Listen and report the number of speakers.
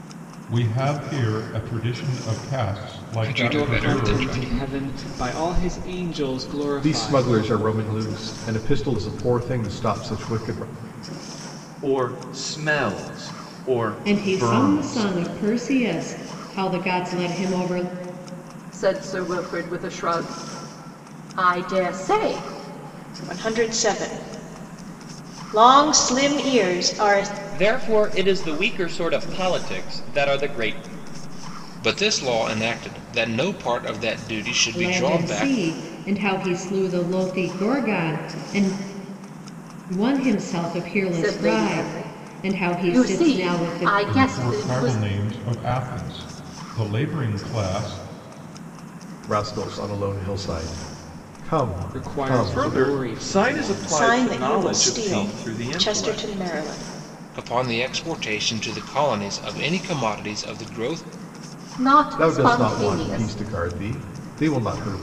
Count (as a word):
ten